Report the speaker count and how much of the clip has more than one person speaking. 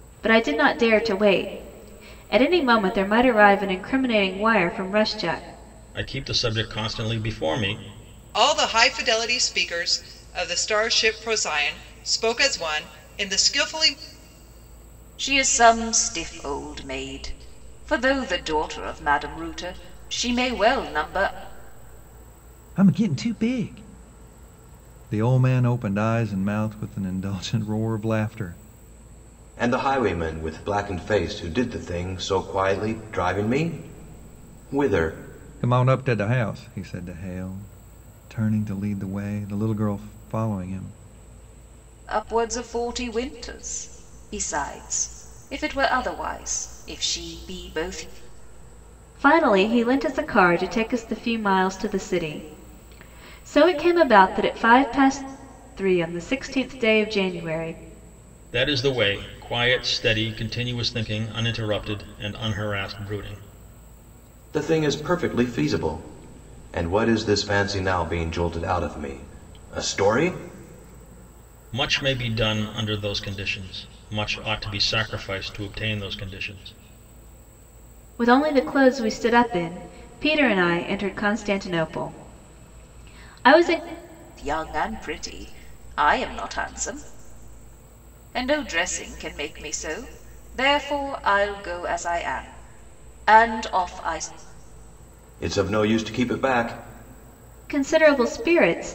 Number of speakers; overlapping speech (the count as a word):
six, no overlap